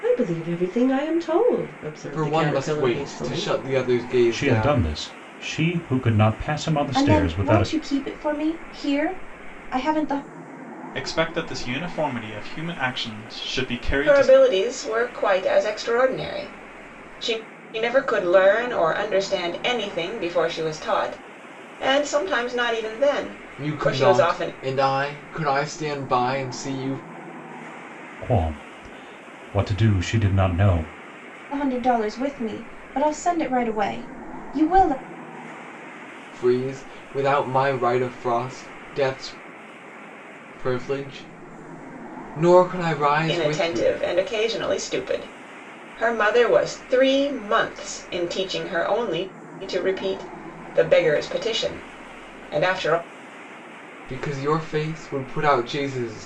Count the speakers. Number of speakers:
six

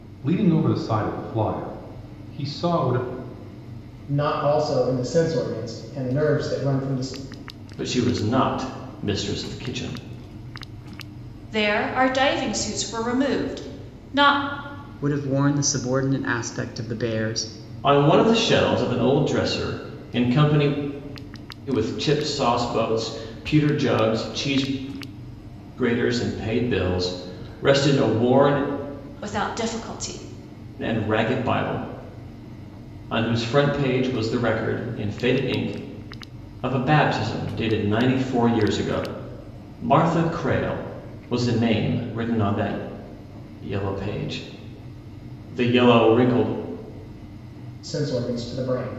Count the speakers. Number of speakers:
five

